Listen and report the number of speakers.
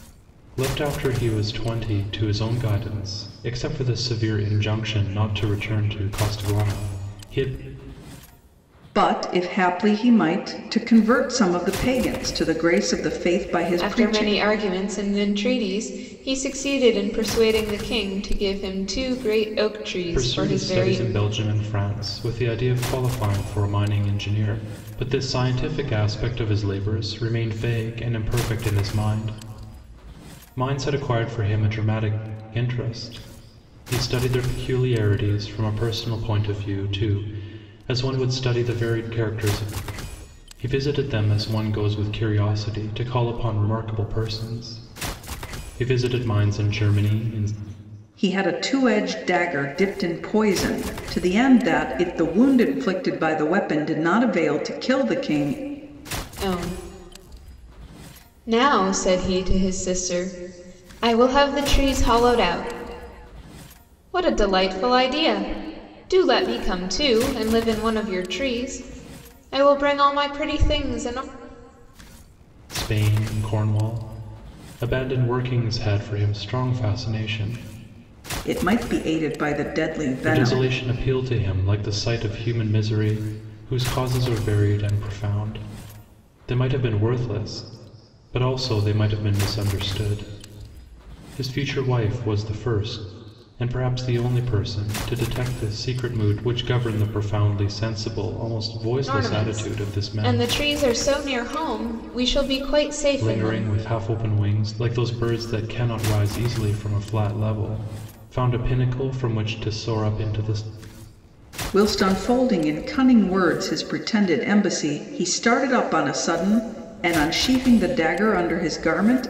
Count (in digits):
3